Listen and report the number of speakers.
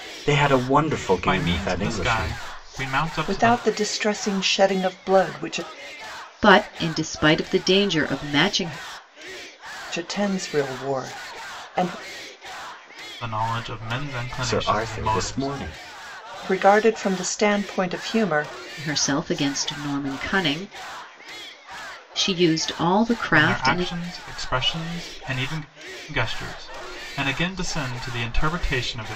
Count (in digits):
4